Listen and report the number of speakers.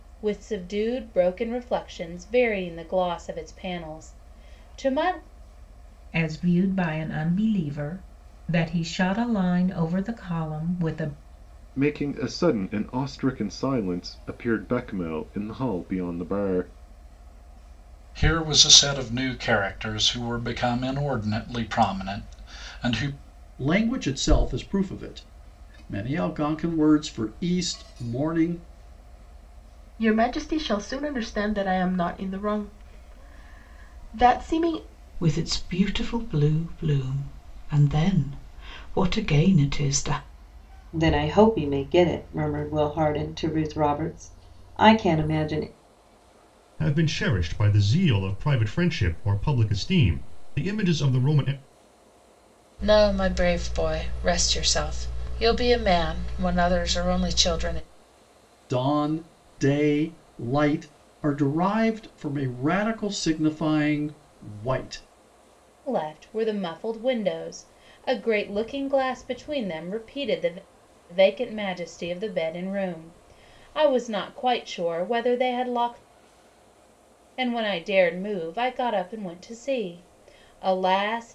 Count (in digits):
10